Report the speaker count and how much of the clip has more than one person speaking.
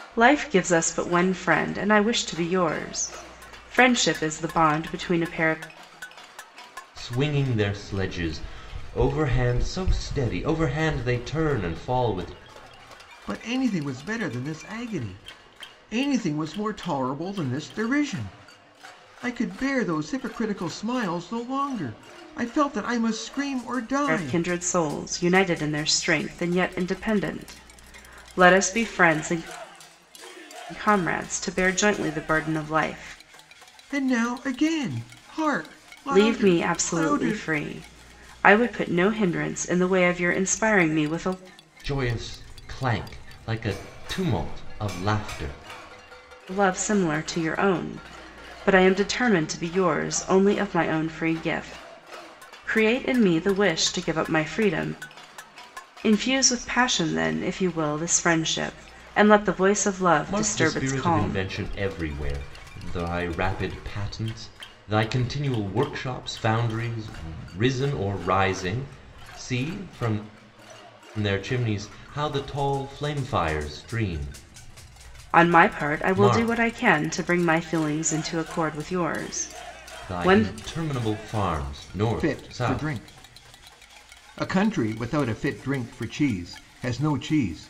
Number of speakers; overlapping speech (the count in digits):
3, about 6%